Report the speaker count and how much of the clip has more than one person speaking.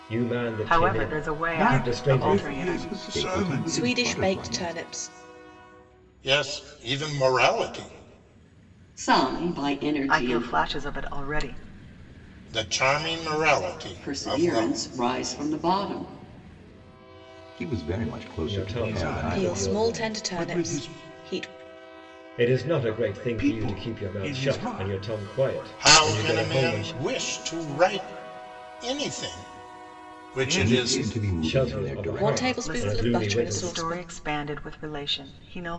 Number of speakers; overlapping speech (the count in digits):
7, about 43%